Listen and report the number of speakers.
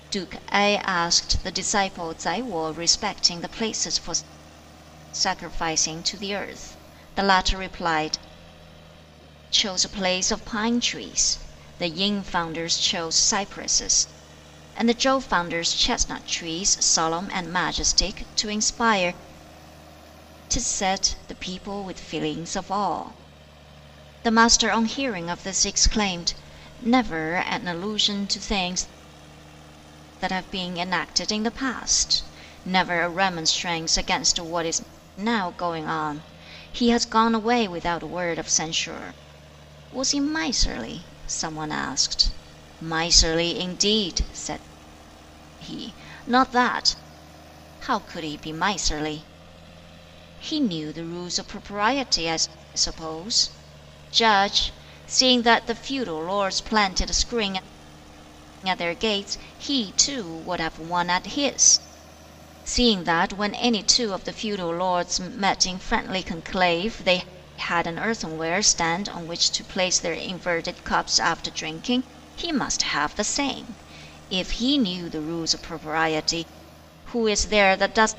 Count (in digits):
1